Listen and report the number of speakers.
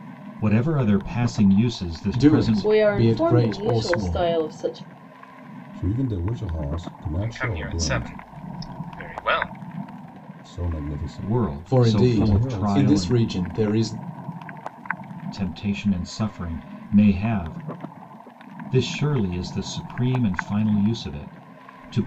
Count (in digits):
5